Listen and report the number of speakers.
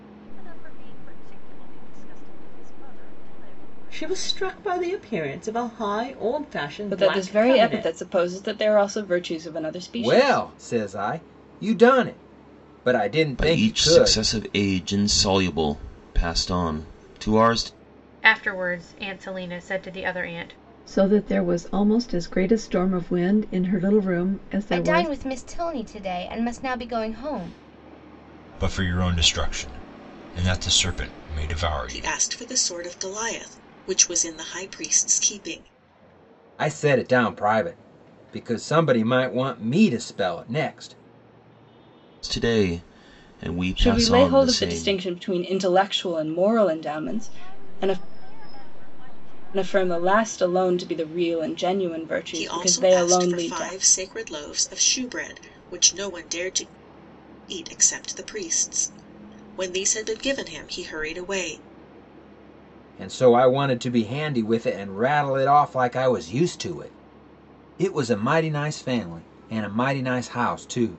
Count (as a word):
ten